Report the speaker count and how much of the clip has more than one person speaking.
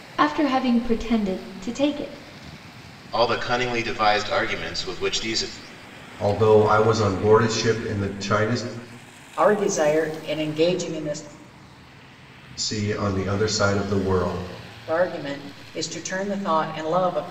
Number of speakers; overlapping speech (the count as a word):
four, no overlap